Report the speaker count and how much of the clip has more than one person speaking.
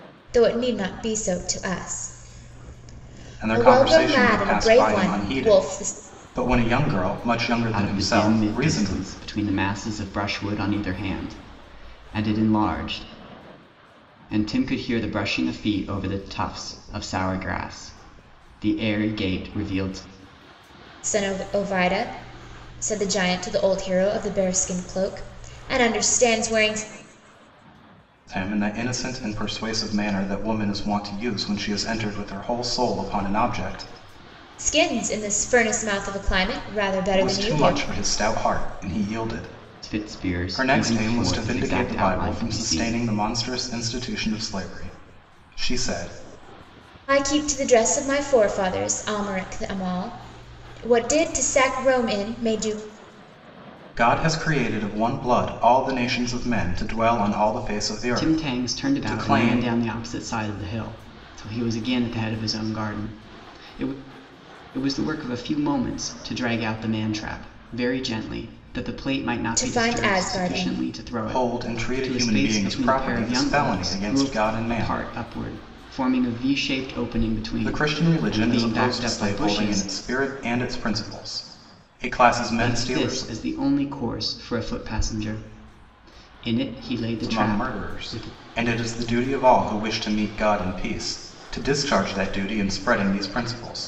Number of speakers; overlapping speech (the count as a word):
three, about 19%